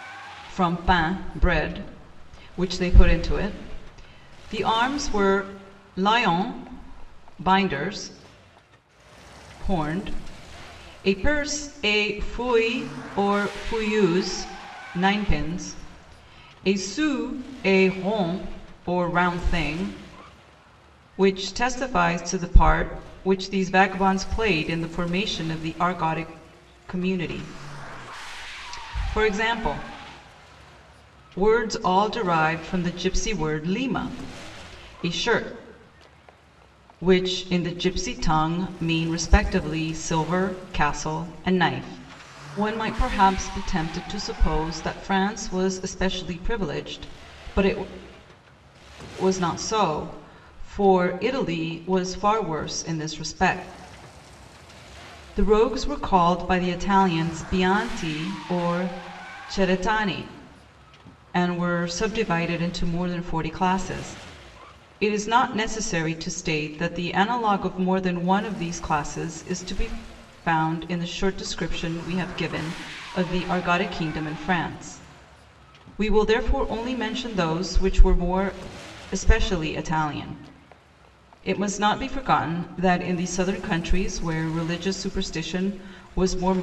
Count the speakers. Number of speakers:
1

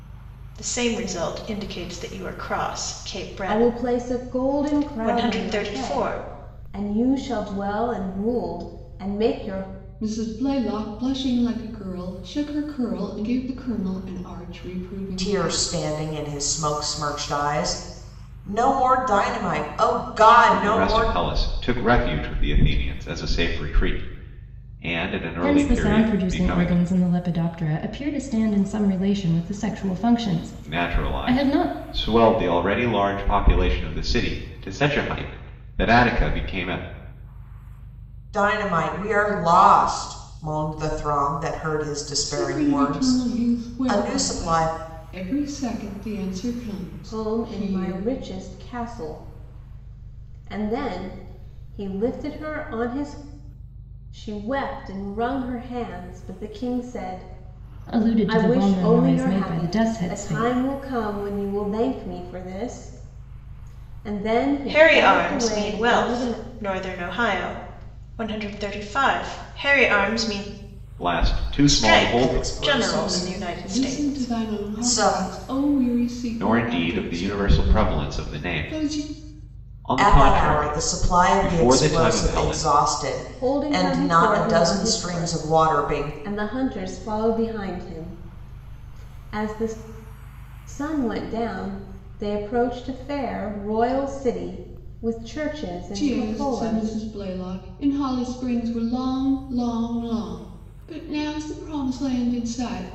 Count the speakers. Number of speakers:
6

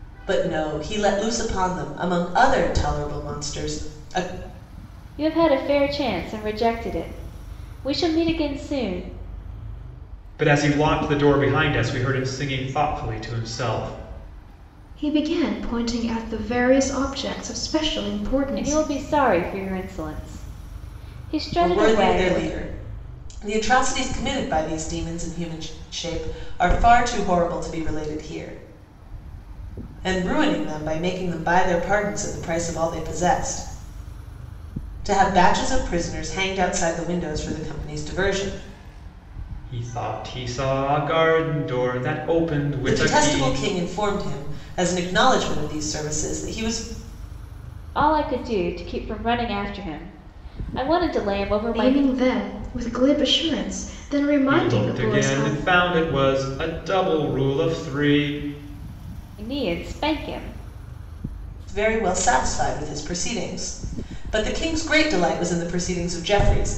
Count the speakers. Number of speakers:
4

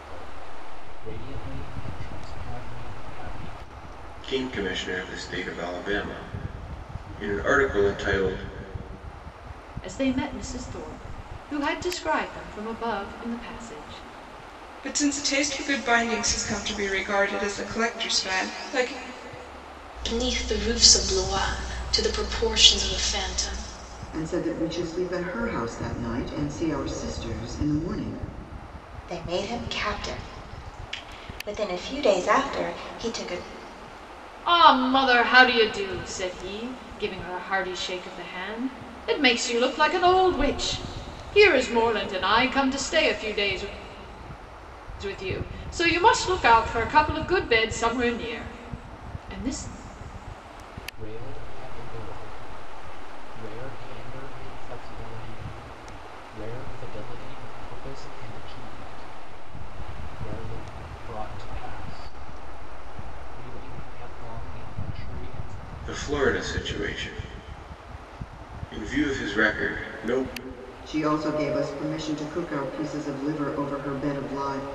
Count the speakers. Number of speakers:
7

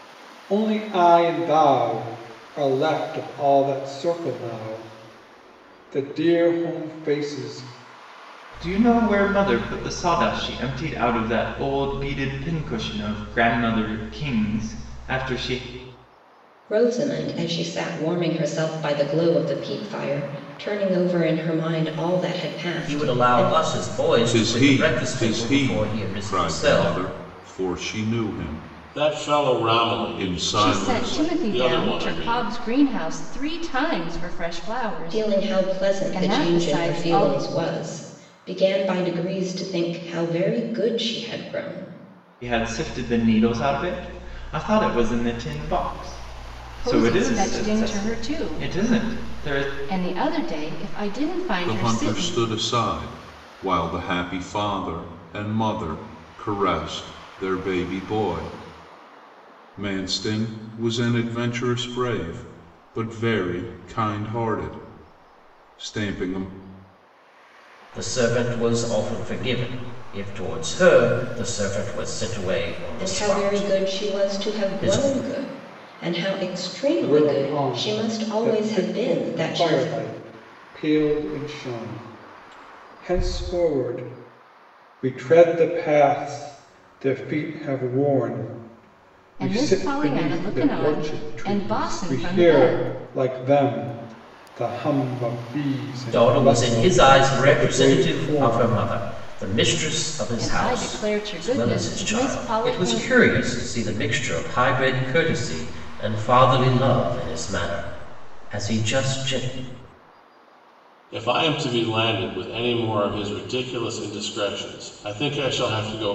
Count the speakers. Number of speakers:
7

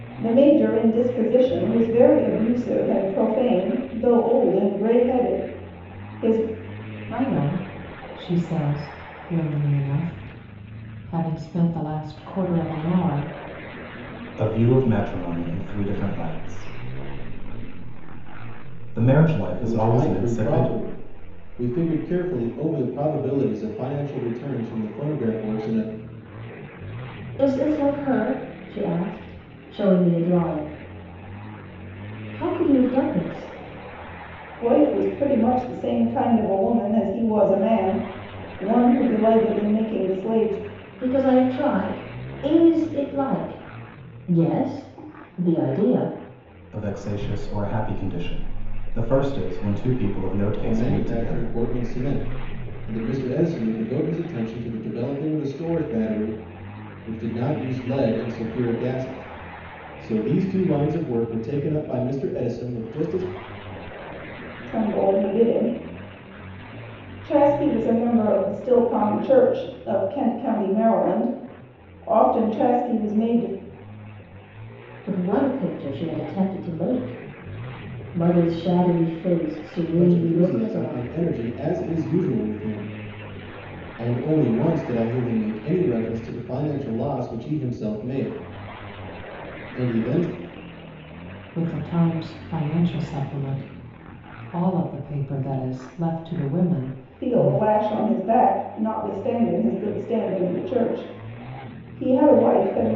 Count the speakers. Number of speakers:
5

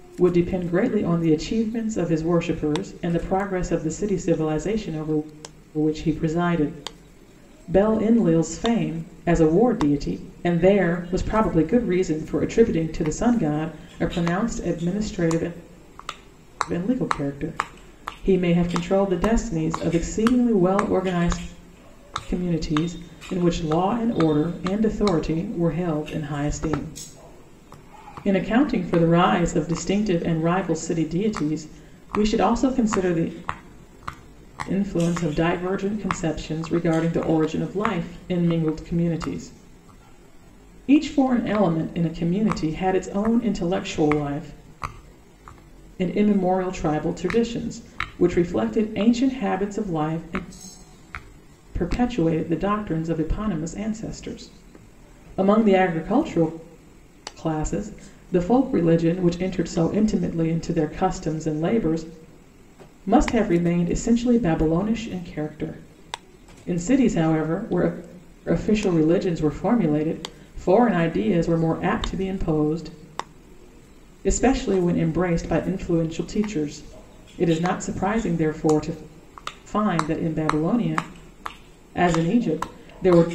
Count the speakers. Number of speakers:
1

